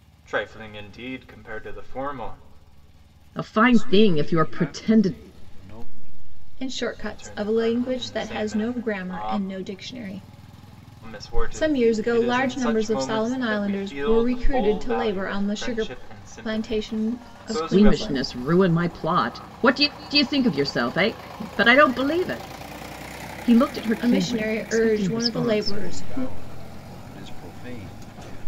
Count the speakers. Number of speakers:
4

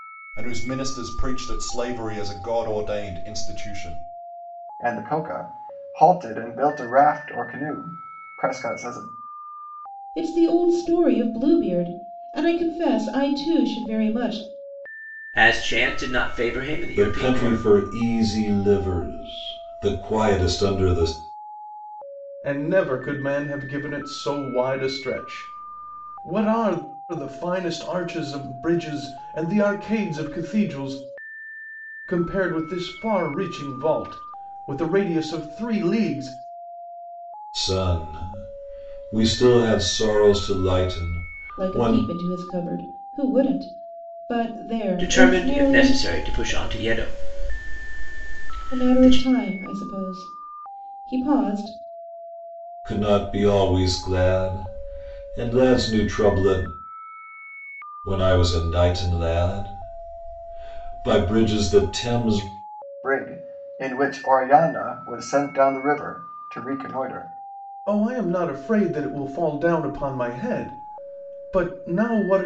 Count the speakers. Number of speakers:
6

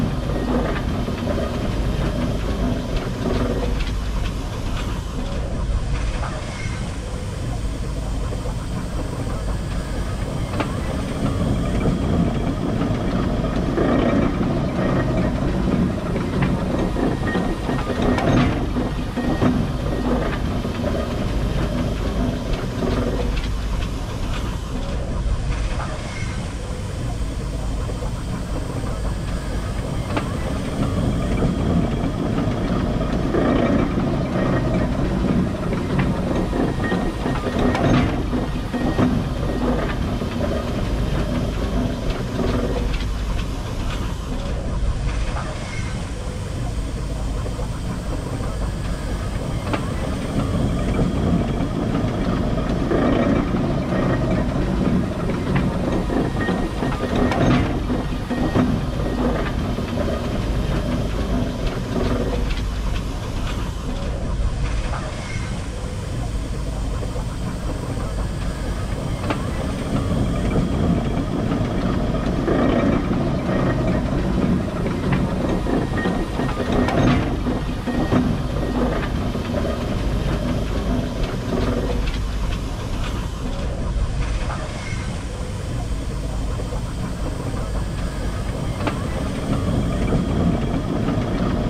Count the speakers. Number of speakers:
0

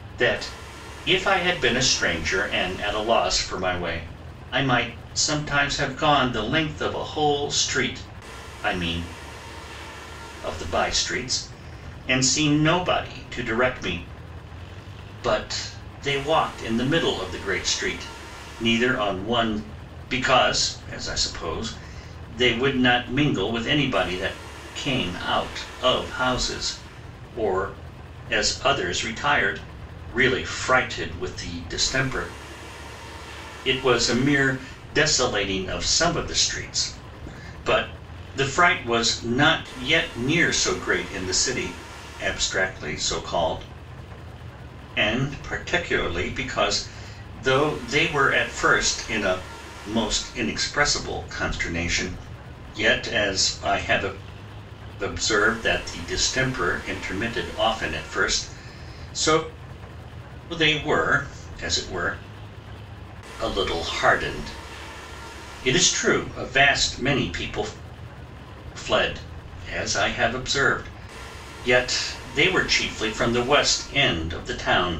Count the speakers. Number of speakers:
1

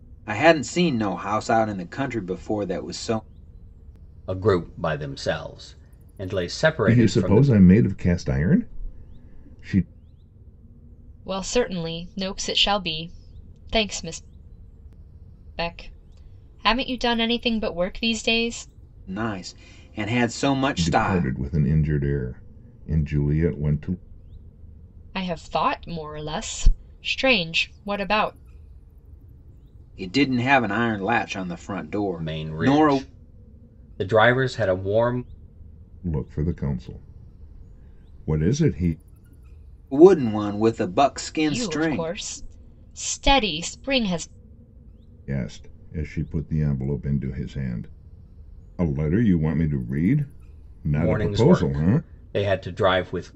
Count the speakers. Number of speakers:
4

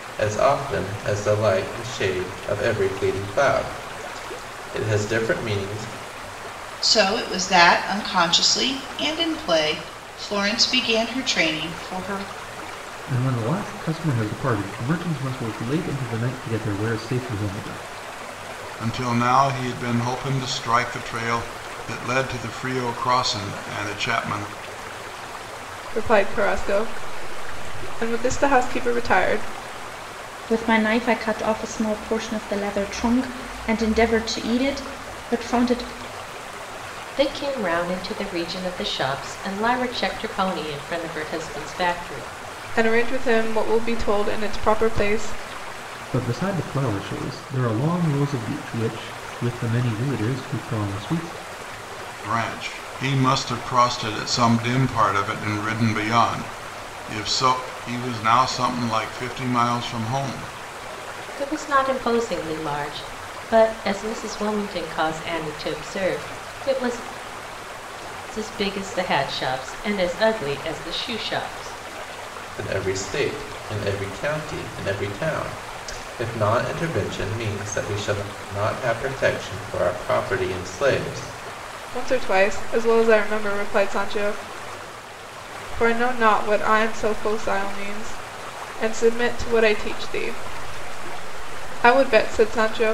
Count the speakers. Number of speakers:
7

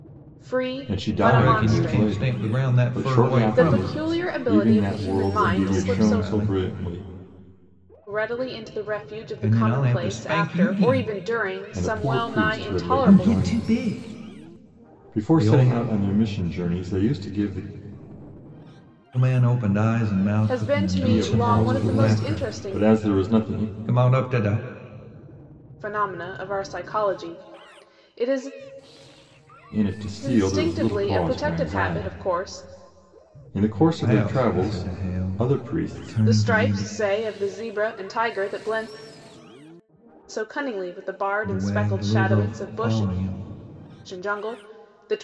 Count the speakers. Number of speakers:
3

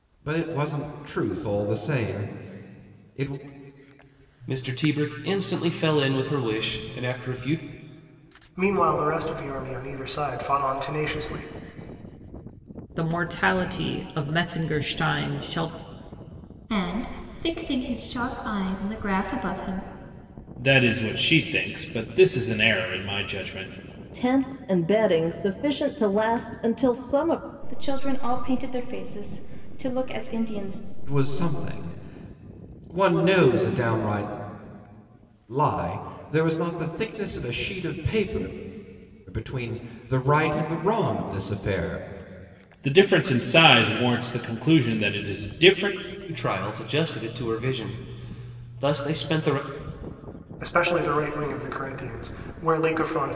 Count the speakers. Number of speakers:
8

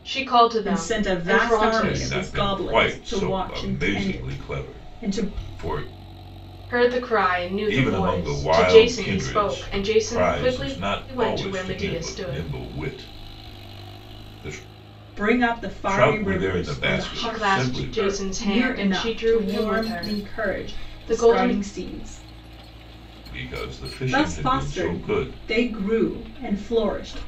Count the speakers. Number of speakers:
3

